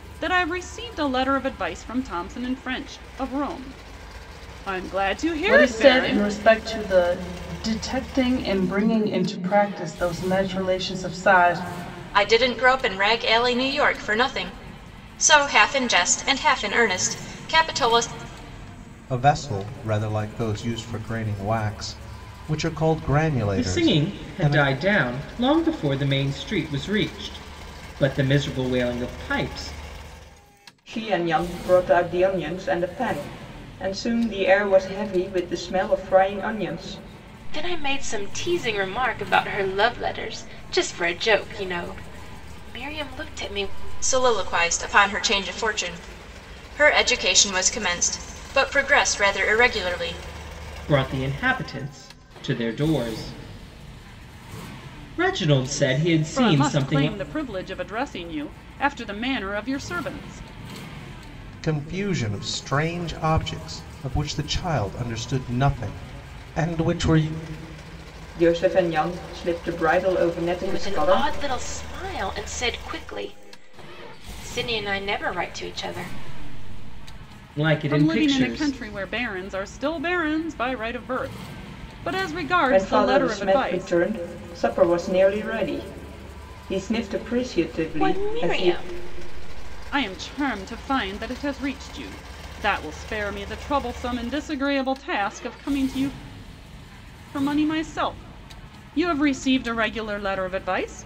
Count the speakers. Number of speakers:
7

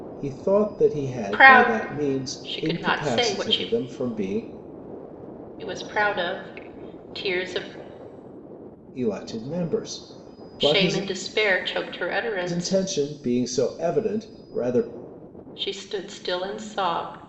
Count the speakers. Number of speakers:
2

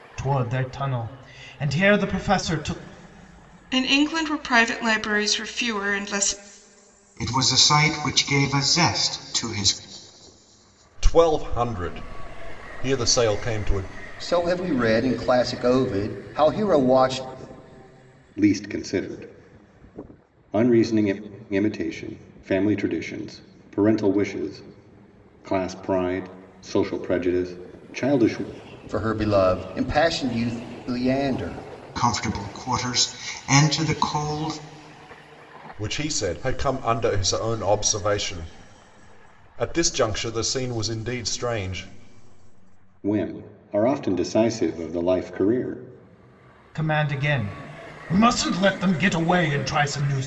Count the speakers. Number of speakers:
6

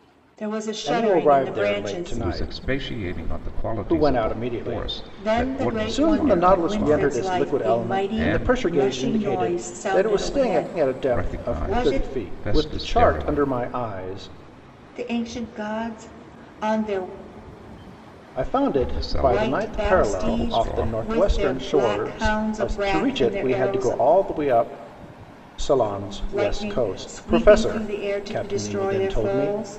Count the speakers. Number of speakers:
3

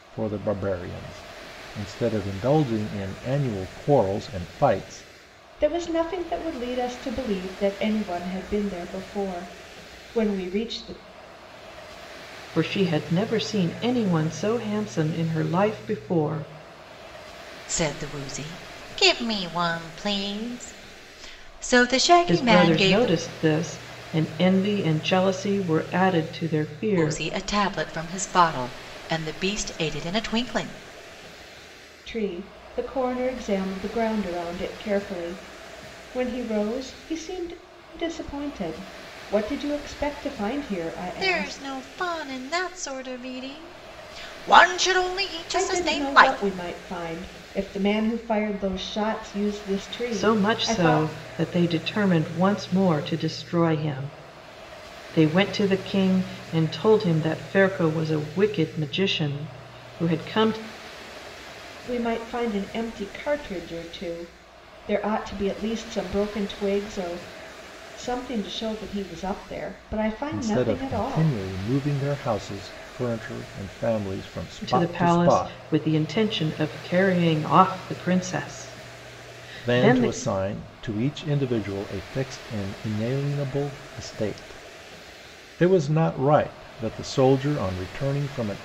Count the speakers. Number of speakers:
4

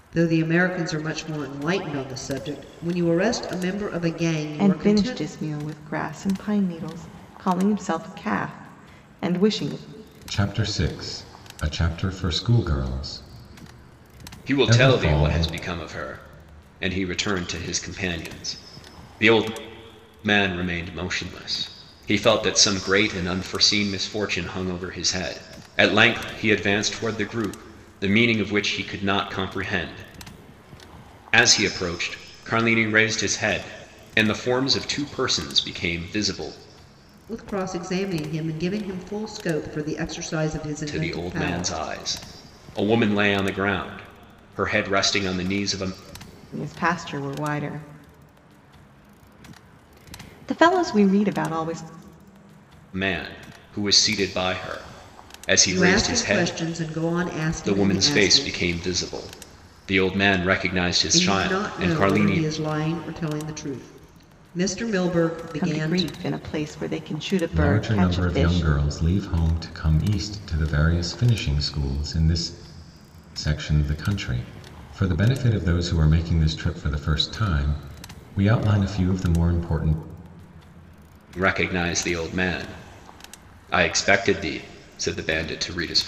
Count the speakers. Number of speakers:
4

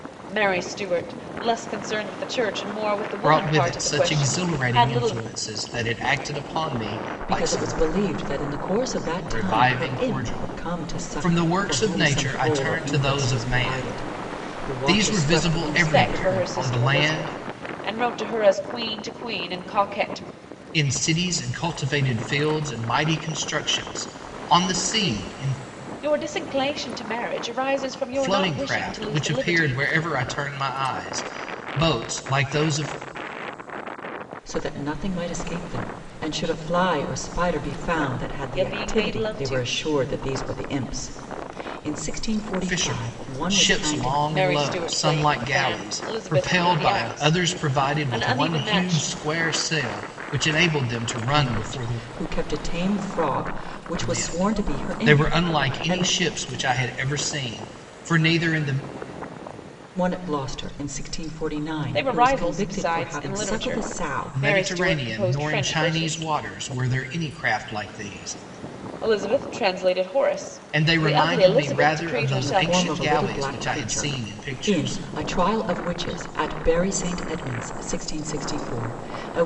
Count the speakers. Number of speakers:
3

